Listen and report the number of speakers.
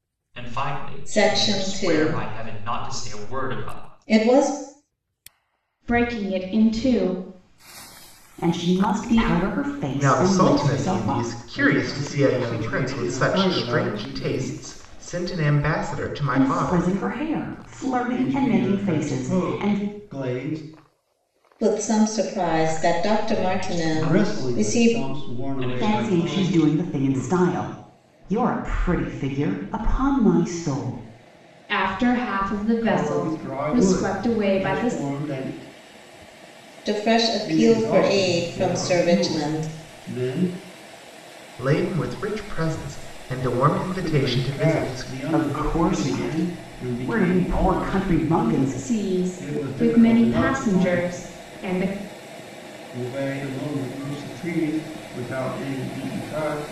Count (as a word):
six